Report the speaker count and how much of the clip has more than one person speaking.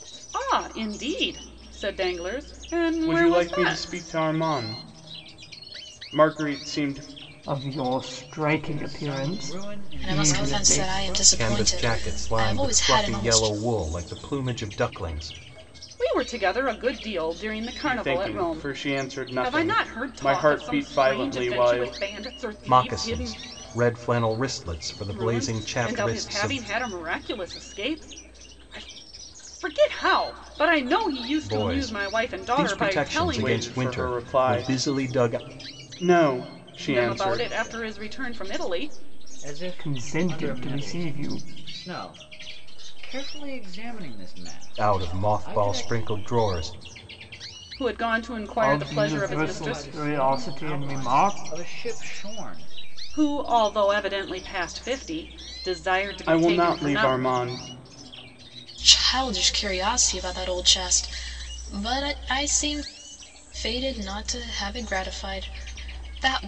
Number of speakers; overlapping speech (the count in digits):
6, about 36%